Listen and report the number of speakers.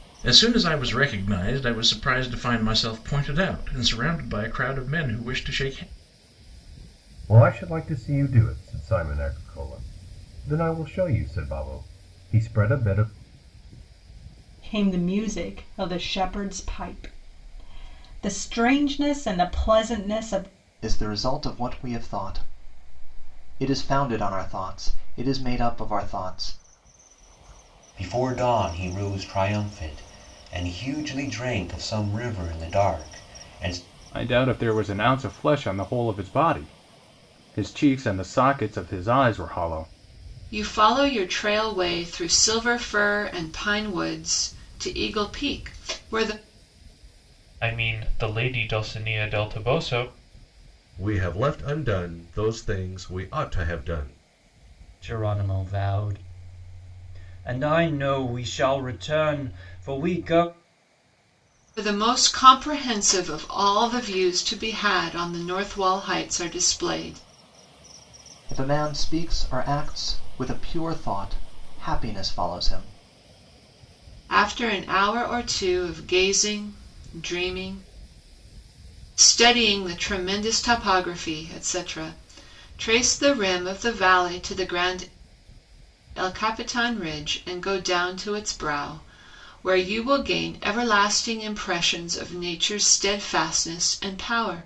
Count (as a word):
ten